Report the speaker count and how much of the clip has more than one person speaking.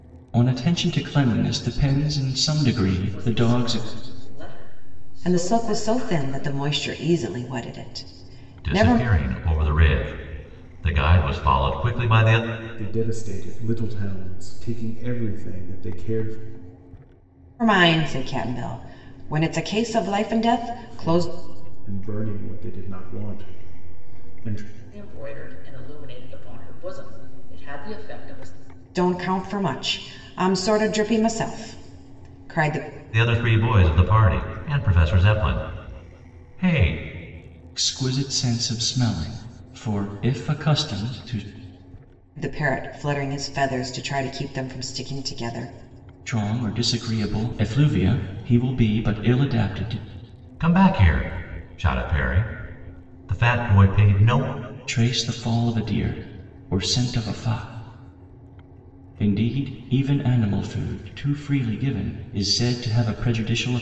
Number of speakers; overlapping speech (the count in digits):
5, about 5%